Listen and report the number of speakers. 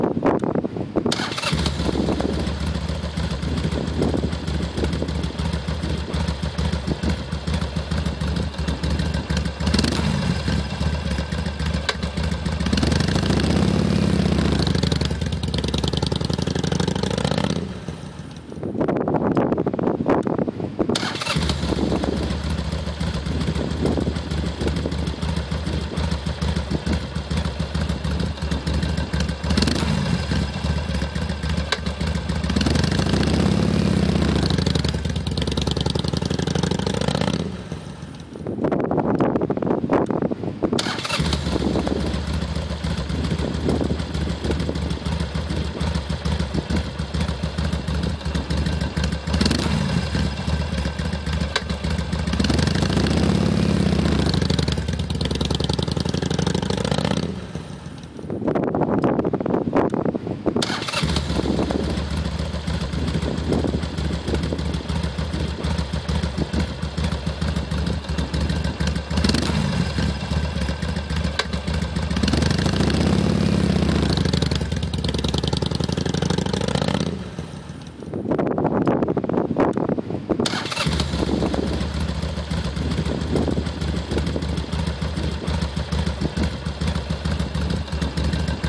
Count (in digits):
0